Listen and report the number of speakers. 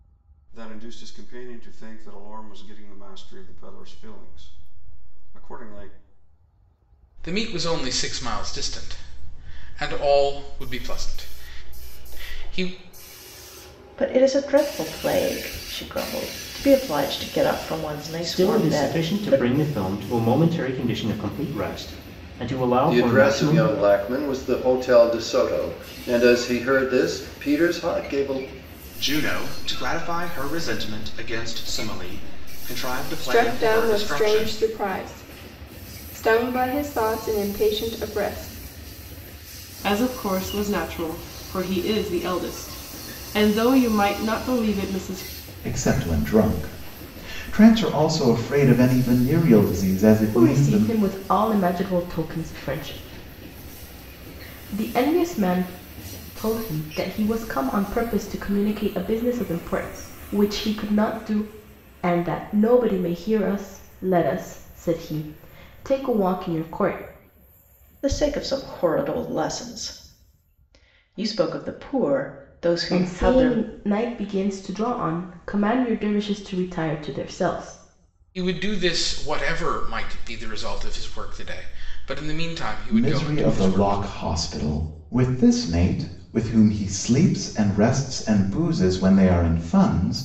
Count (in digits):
10